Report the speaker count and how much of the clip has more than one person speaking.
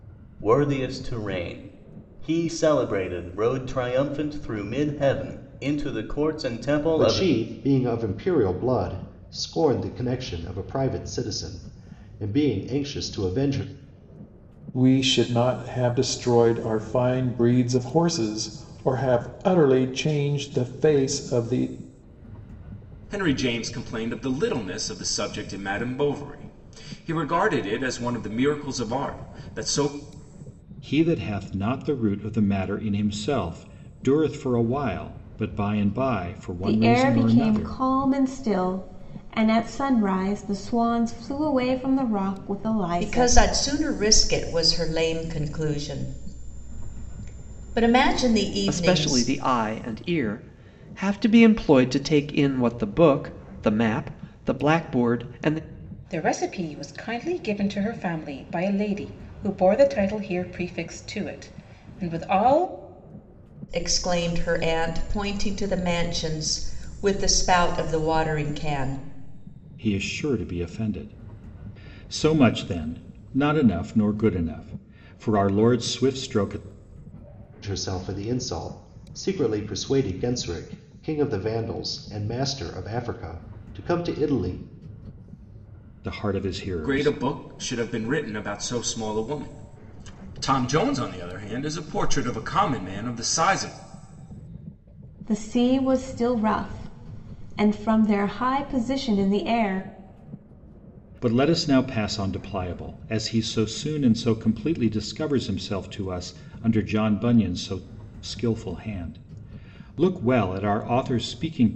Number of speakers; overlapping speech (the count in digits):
9, about 3%